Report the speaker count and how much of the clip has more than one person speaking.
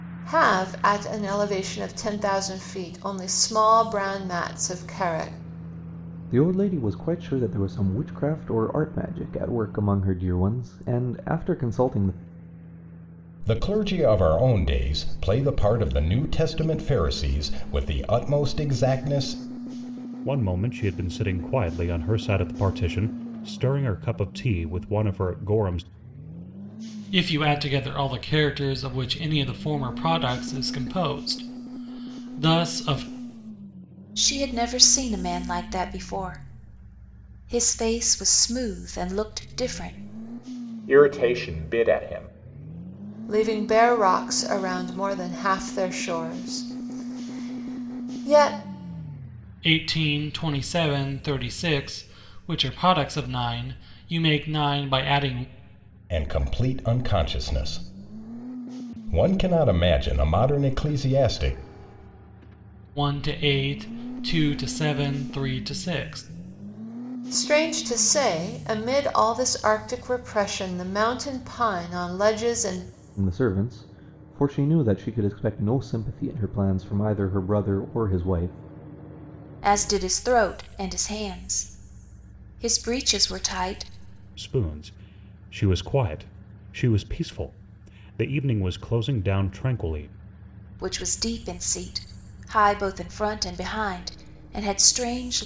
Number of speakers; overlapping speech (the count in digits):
7, no overlap